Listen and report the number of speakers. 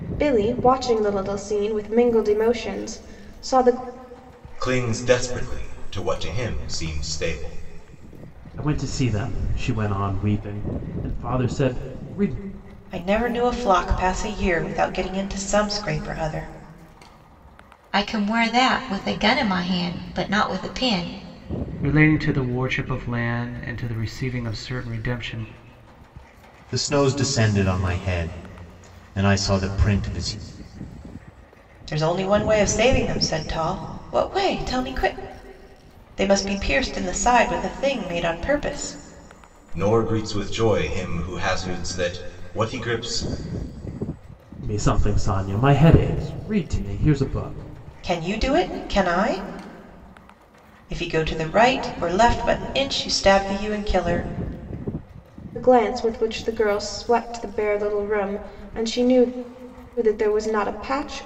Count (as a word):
seven